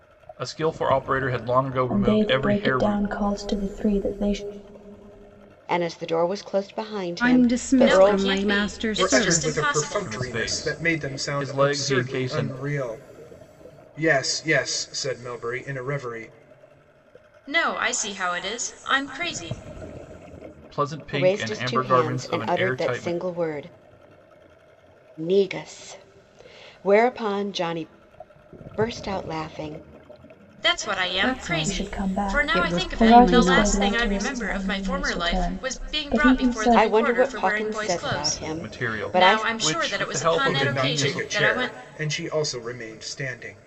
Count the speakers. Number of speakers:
6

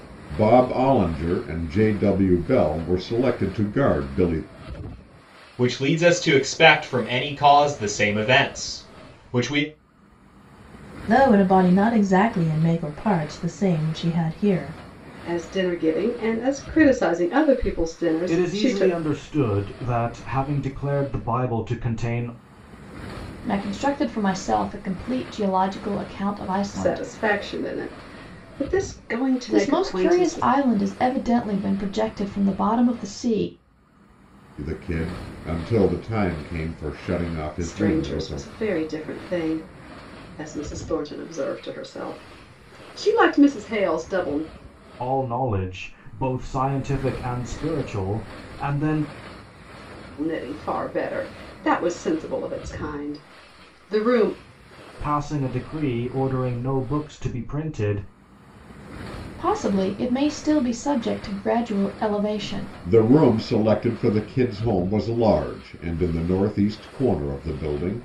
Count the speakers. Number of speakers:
6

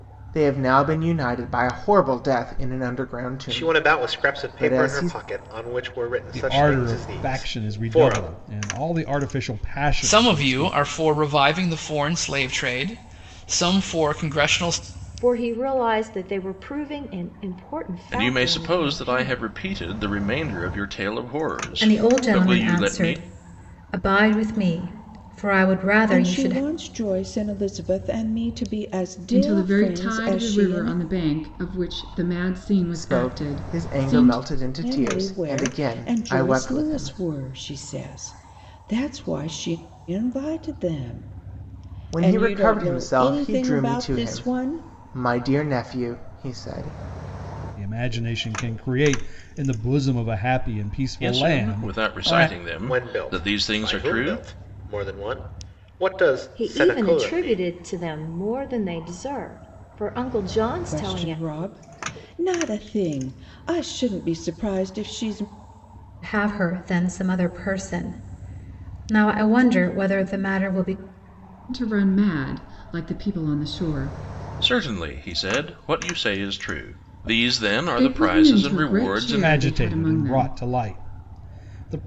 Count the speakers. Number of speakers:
9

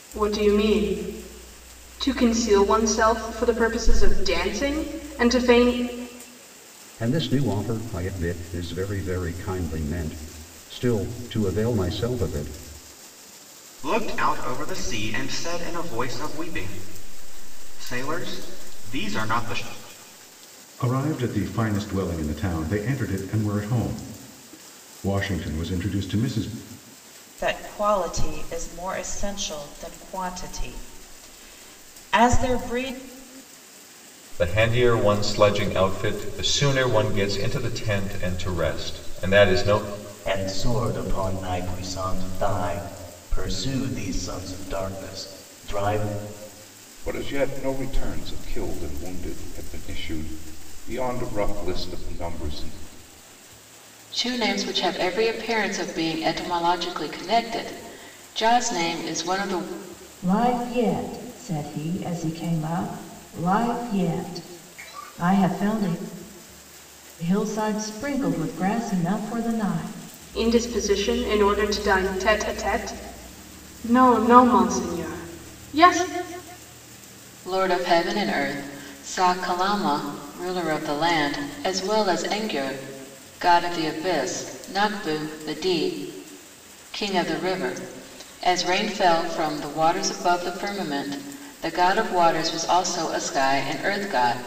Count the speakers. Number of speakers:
10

